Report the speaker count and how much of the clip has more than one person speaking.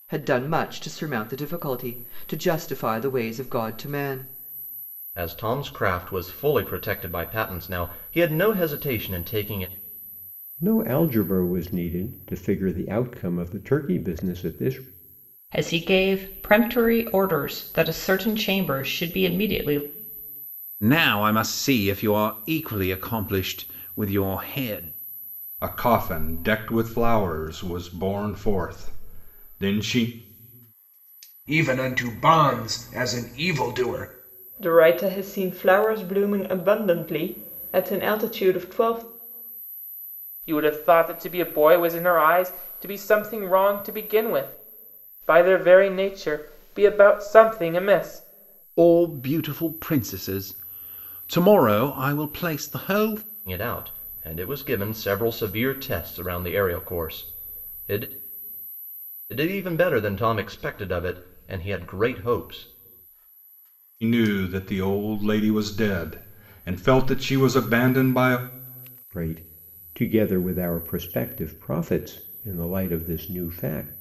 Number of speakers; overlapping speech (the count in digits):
9, no overlap